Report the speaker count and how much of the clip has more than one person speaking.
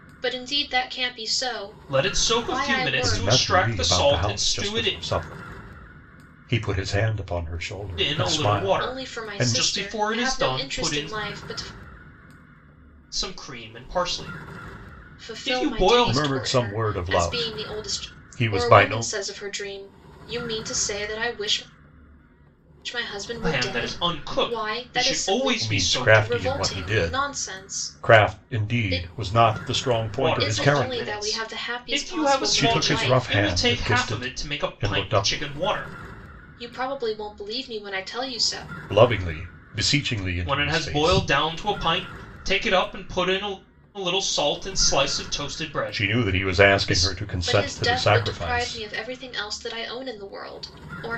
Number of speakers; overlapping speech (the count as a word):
three, about 46%